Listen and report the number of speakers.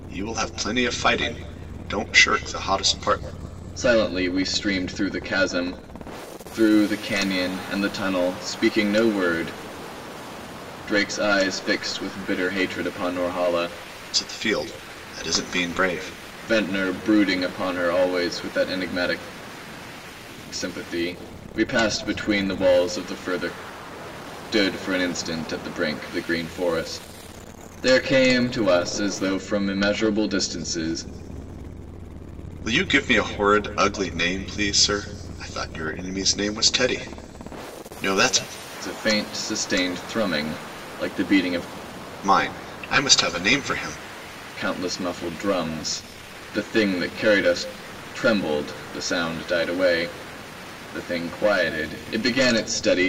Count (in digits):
2